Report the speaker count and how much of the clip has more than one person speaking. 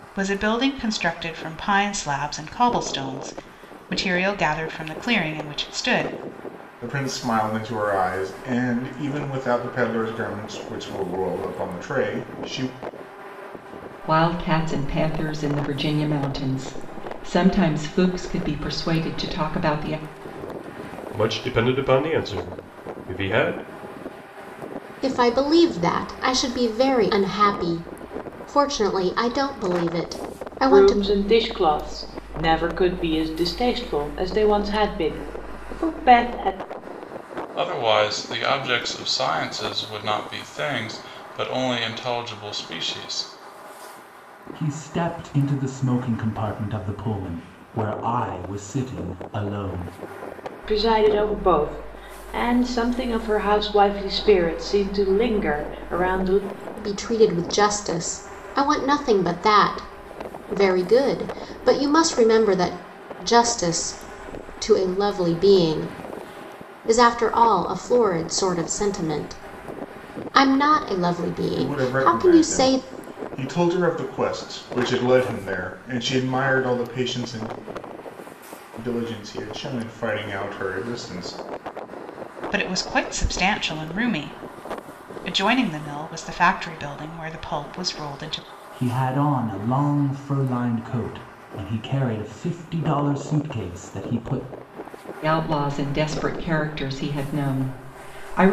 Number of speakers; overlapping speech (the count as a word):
eight, about 2%